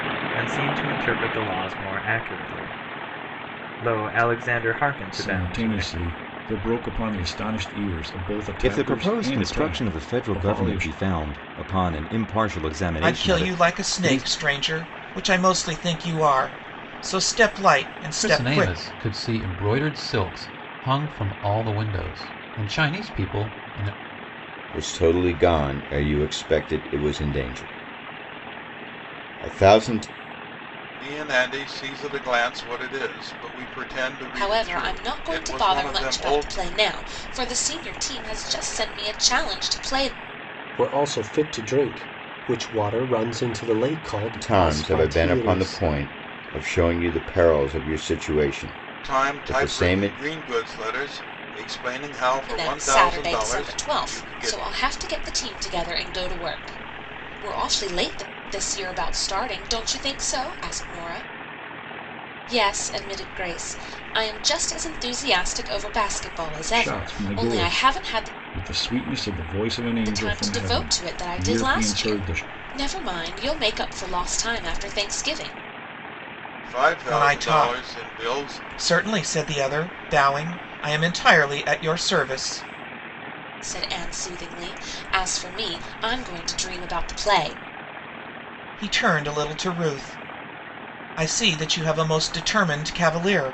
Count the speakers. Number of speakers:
9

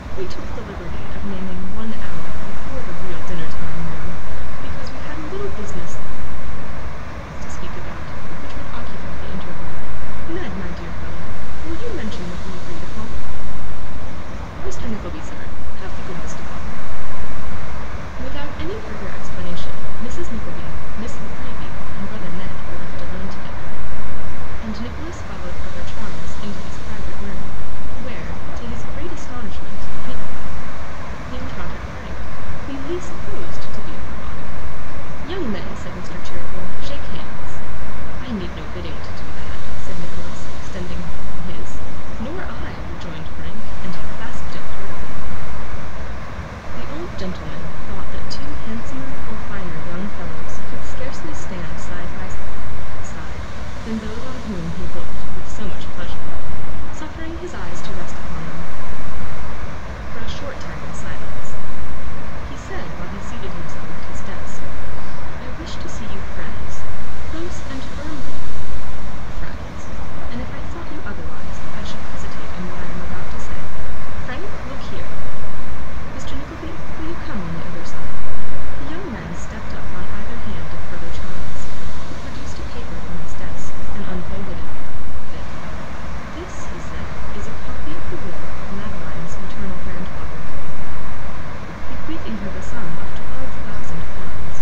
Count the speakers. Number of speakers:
1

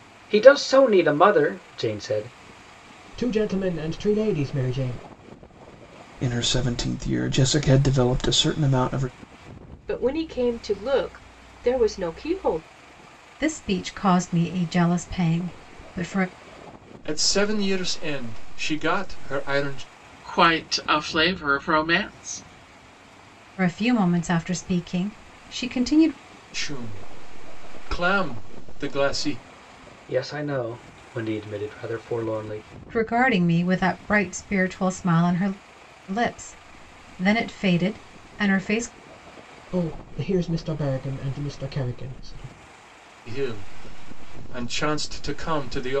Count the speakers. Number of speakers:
7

